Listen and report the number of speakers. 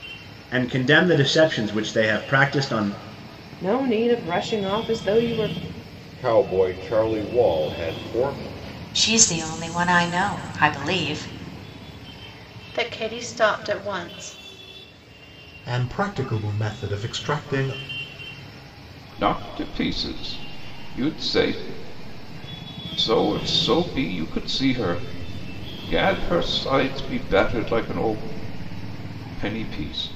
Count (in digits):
7